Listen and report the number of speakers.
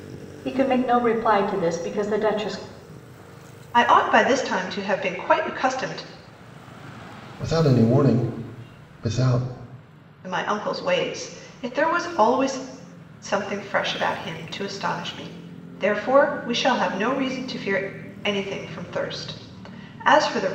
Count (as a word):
three